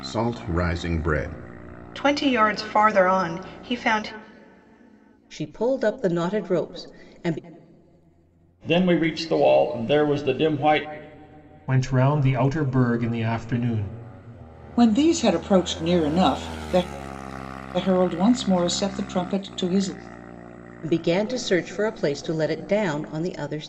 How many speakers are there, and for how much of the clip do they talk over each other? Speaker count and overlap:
6, no overlap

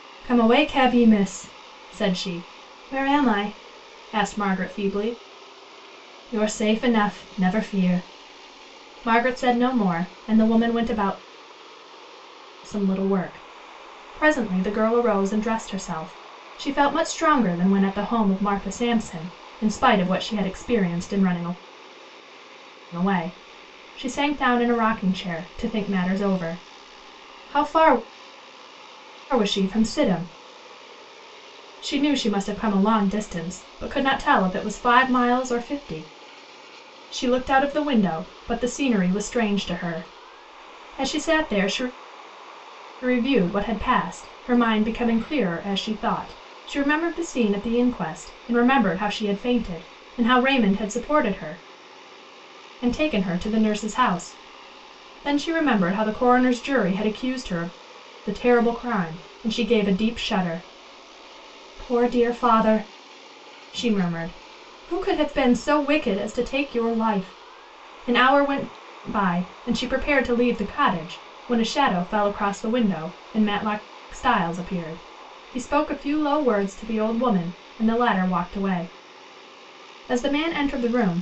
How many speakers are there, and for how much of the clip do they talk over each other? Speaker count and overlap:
1, no overlap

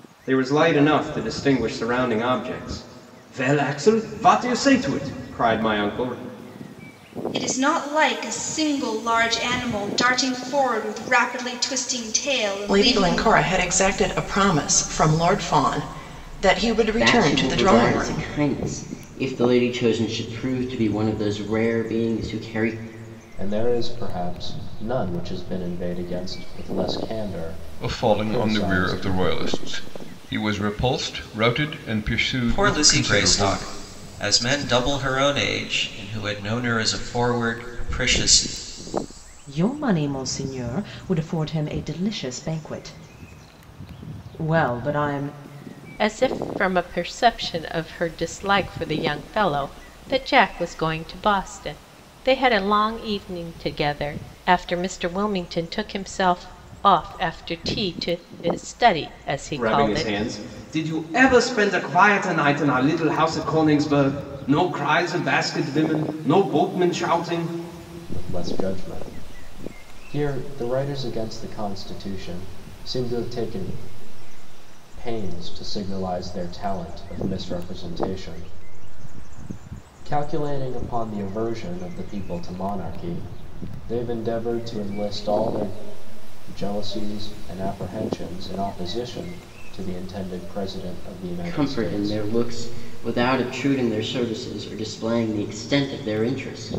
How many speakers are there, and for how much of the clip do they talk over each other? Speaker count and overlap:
9, about 6%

